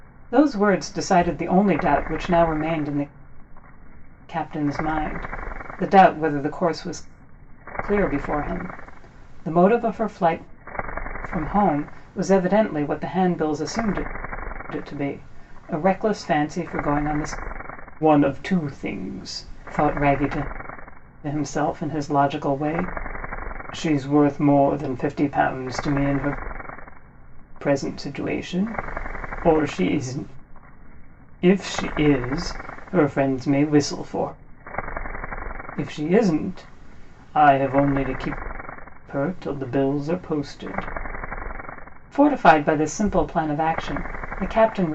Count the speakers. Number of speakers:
1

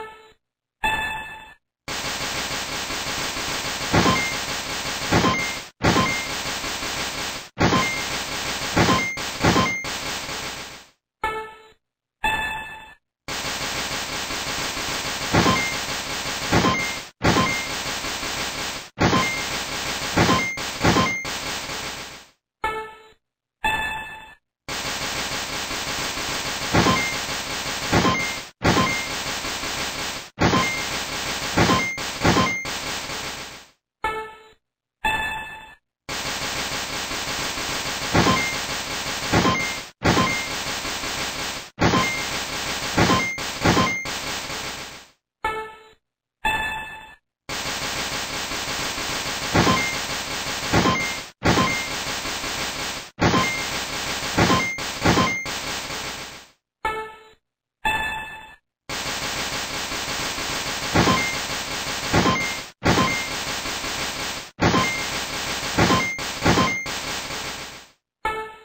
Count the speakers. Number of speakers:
0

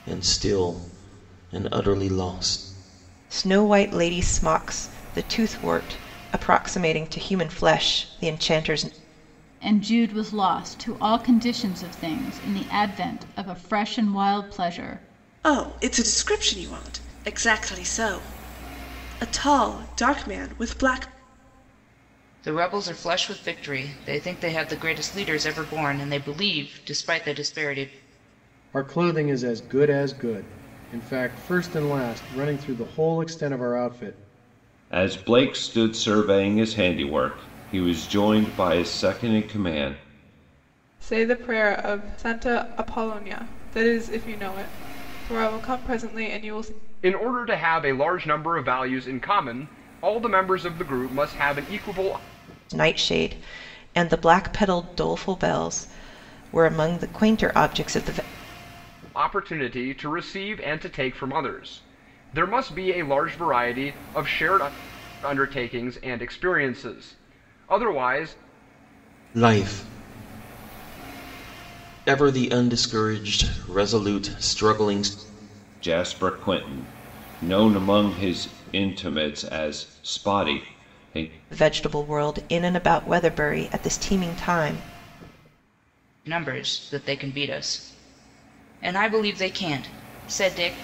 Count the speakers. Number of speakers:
9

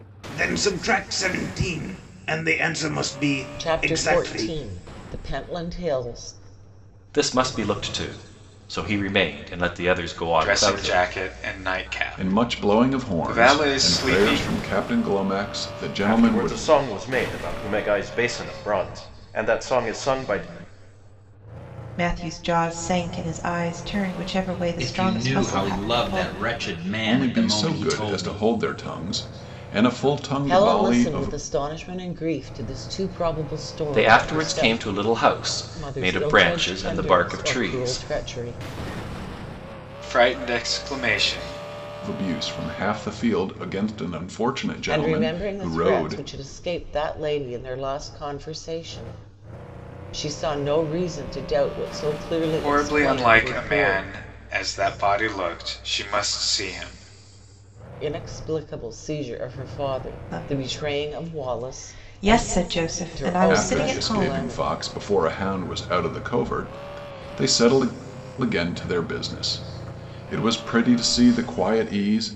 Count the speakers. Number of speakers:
8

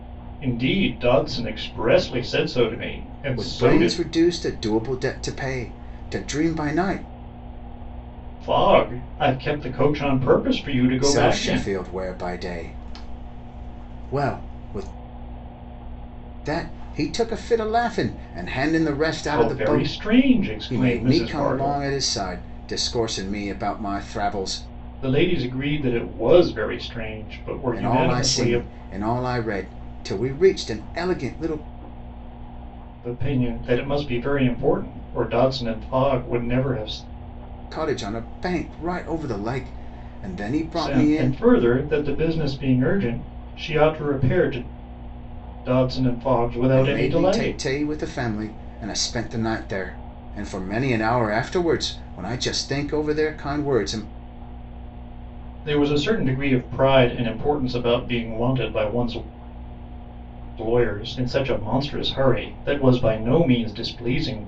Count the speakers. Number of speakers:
2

